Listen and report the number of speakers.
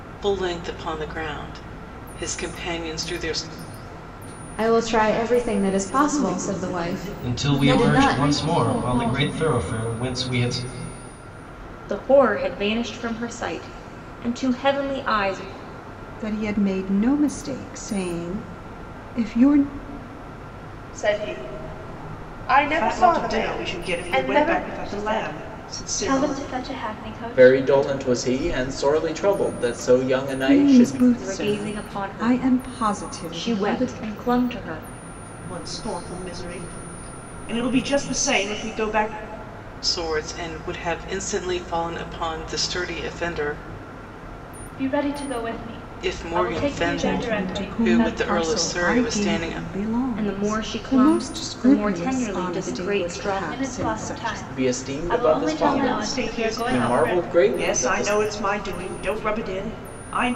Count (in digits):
10